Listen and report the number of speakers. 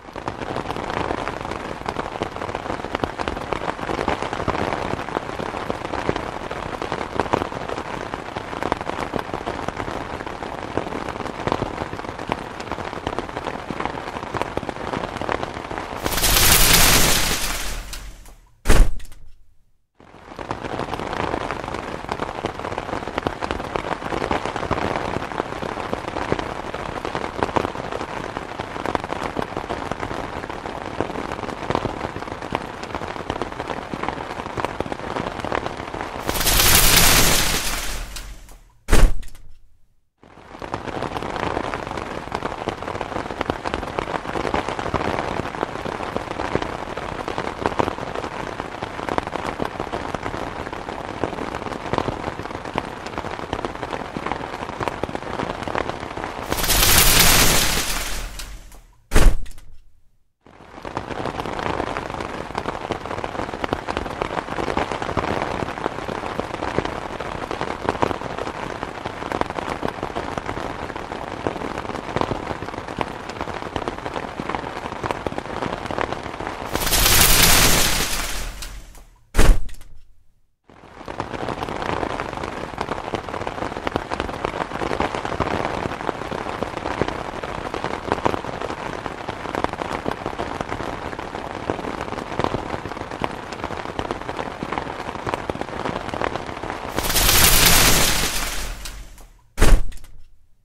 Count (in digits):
0